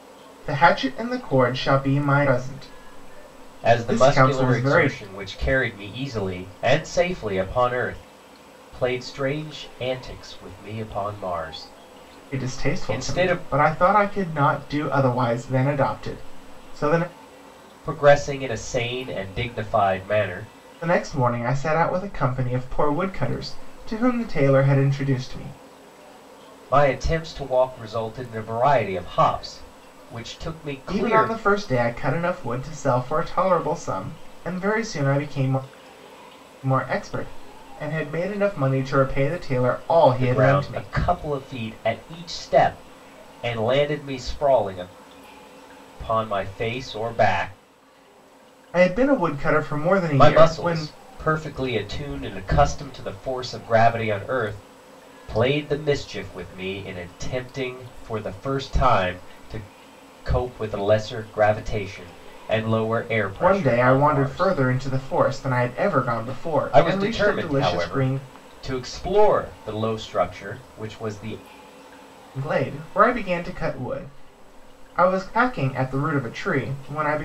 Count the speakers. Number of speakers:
two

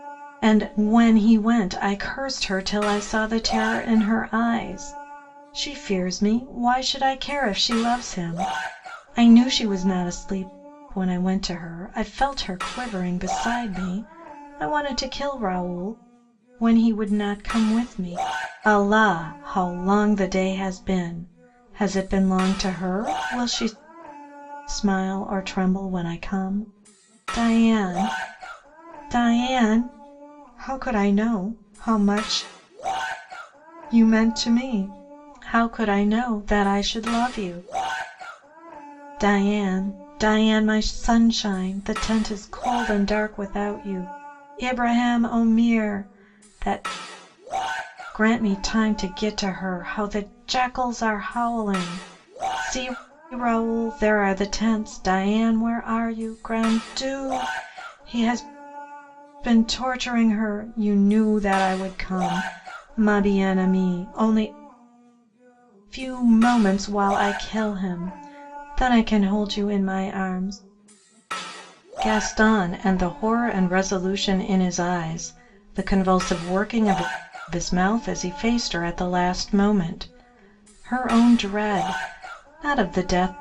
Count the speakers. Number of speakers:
one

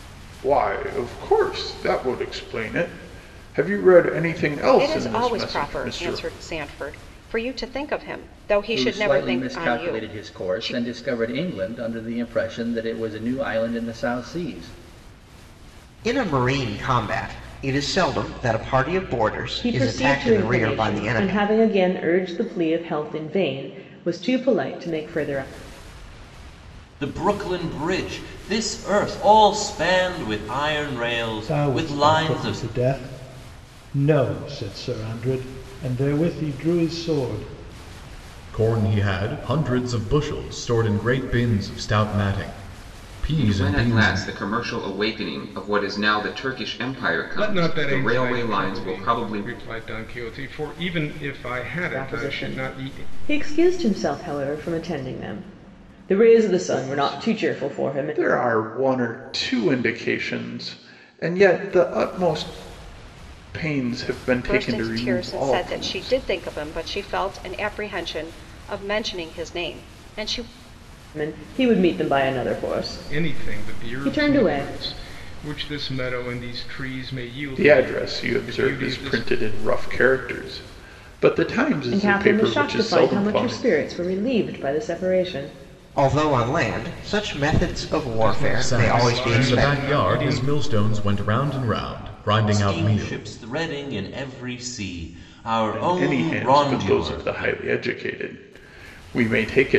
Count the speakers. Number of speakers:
ten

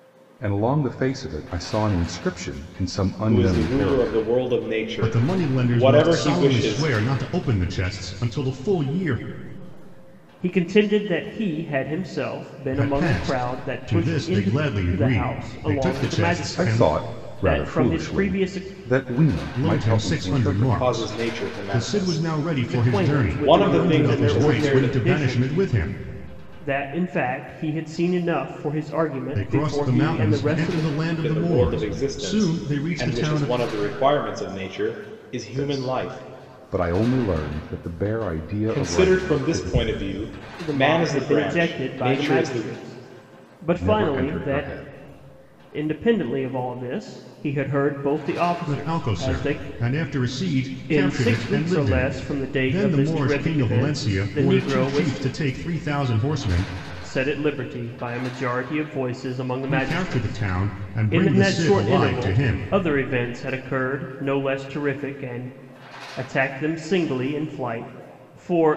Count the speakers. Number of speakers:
four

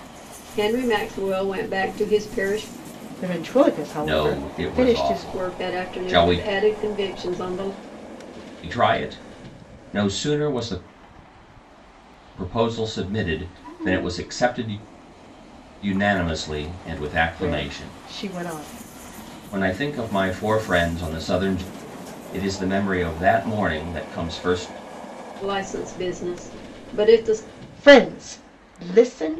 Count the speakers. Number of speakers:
three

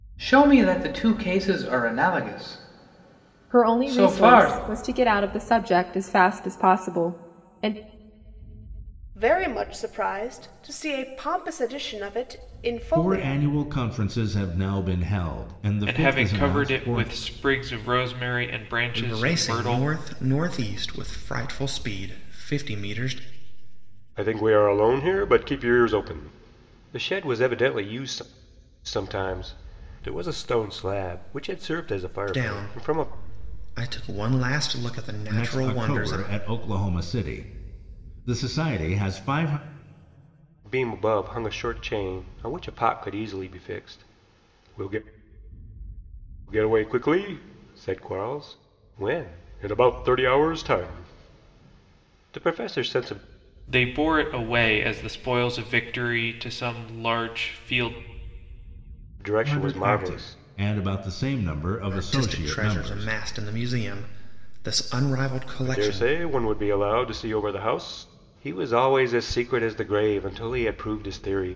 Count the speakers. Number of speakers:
seven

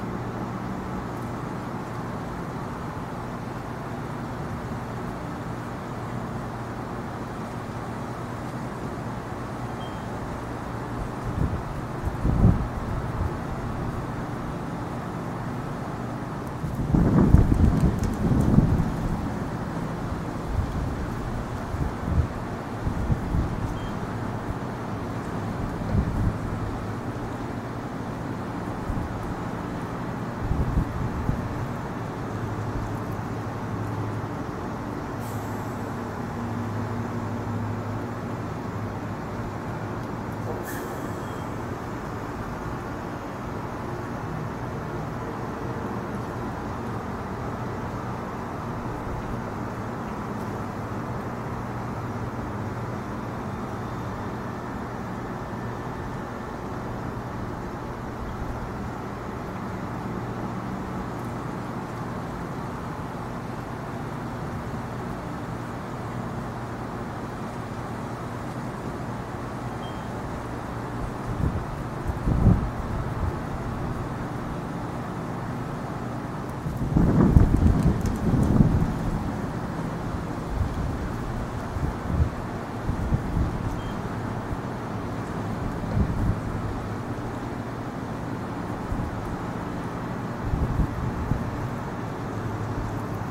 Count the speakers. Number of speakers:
zero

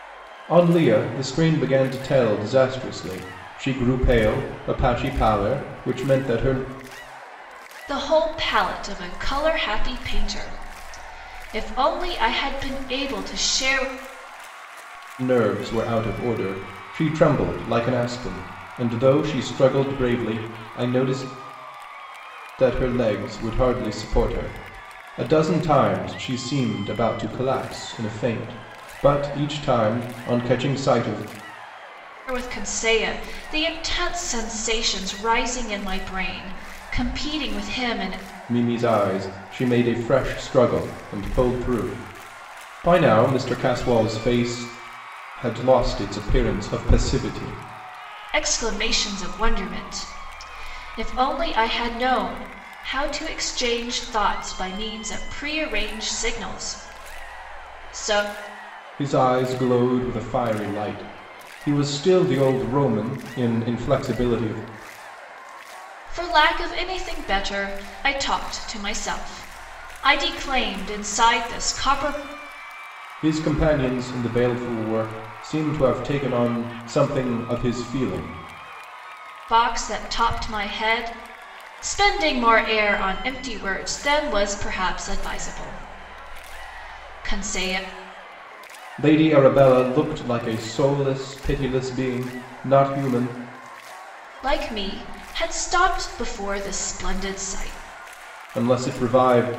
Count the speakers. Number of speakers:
two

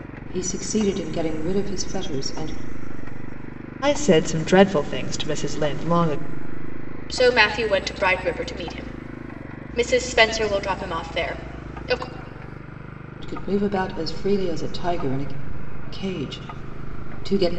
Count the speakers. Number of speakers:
three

